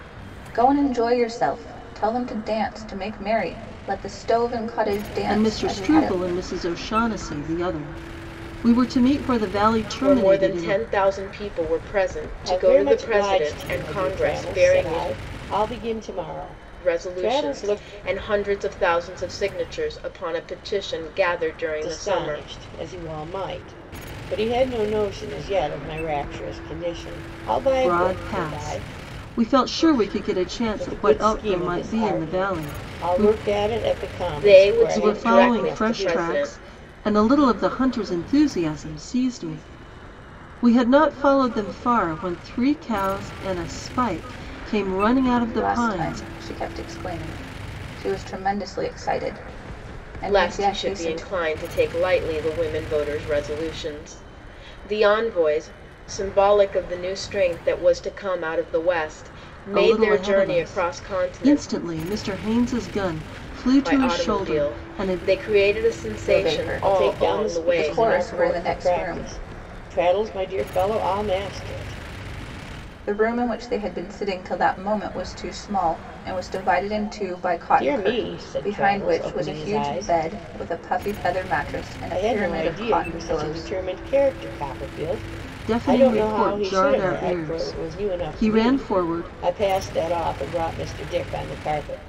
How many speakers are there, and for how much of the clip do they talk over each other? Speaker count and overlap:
four, about 31%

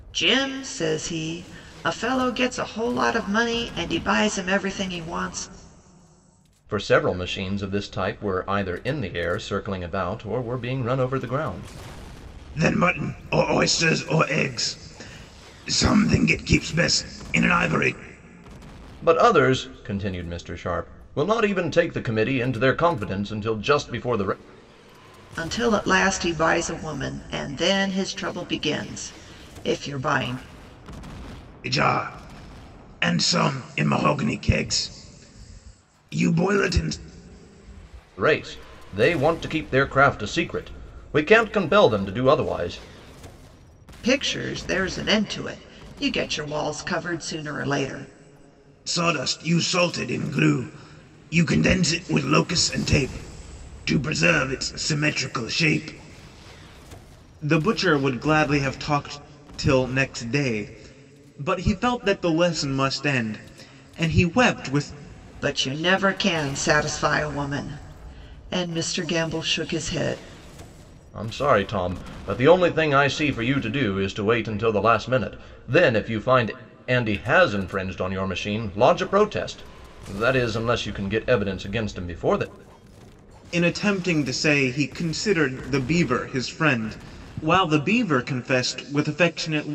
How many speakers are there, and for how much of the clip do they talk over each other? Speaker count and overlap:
three, no overlap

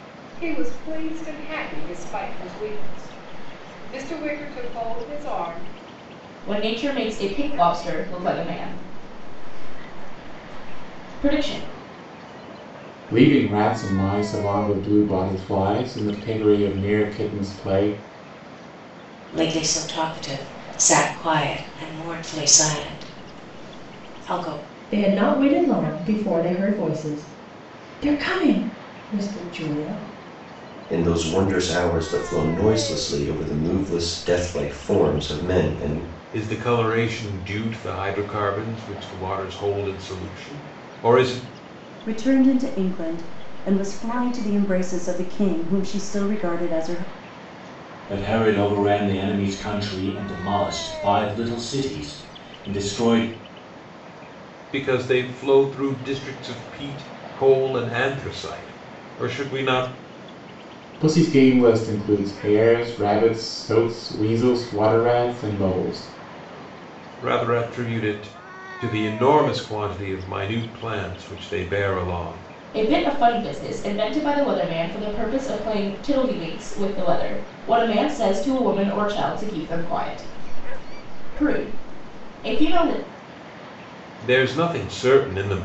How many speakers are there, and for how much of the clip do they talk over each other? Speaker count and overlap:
nine, no overlap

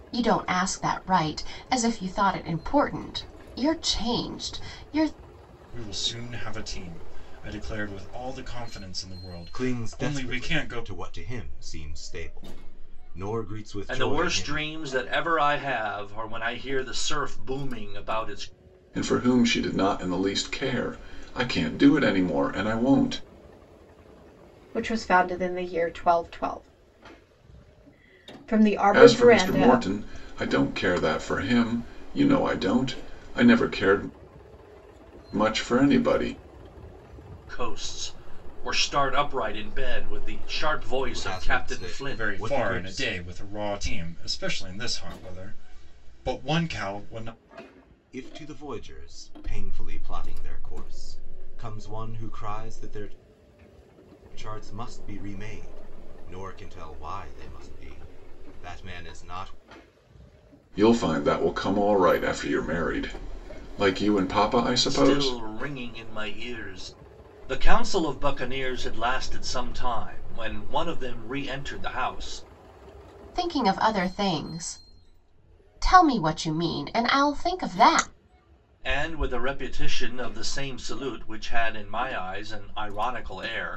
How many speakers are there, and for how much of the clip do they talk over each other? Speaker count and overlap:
six, about 7%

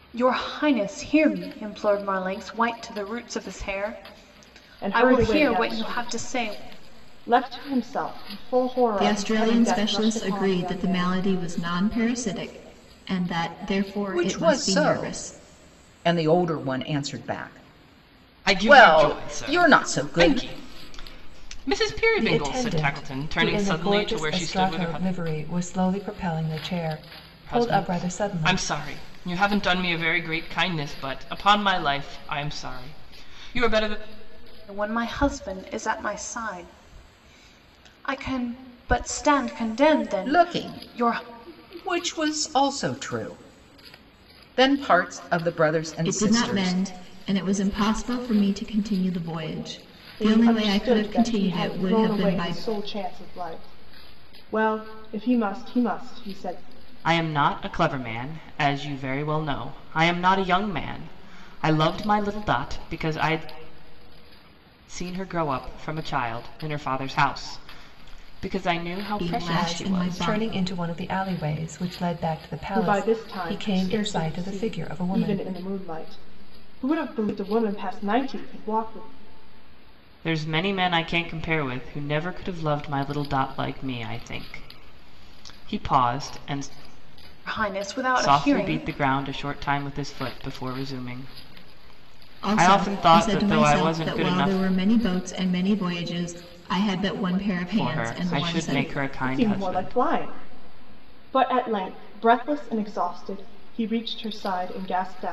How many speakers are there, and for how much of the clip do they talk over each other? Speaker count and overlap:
six, about 24%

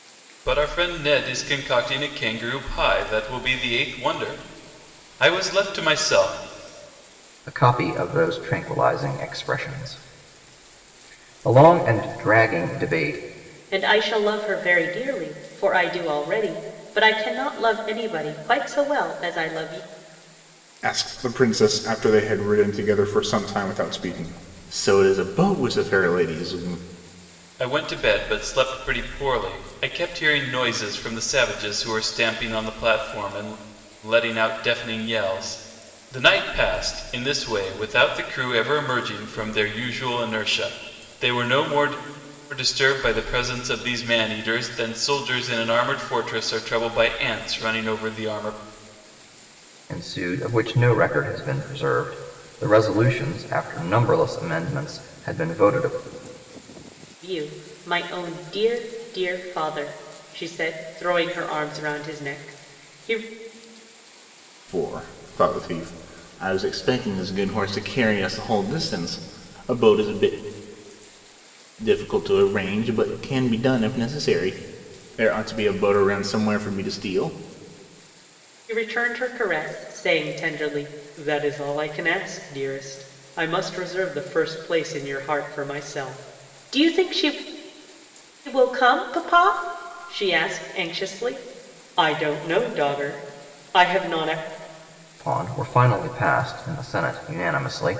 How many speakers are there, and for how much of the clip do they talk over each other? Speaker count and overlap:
four, no overlap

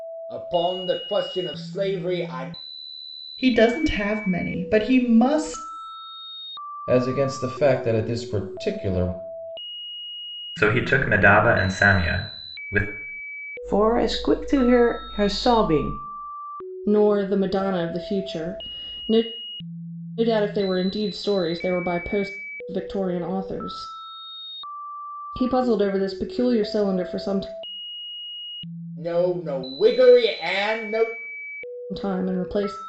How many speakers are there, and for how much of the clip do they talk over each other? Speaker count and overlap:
six, no overlap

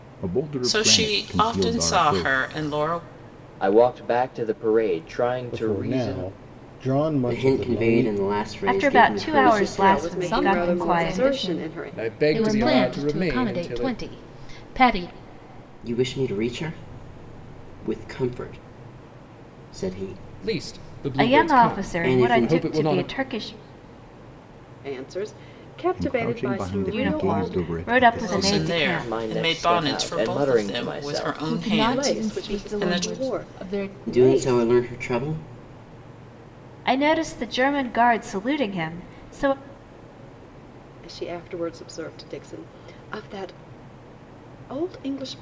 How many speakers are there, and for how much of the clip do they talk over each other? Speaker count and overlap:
ten, about 45%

